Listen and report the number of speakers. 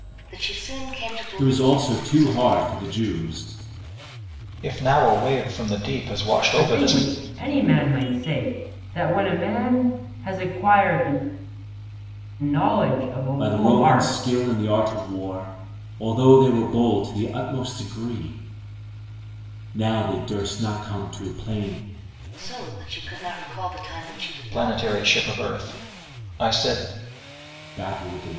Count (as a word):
four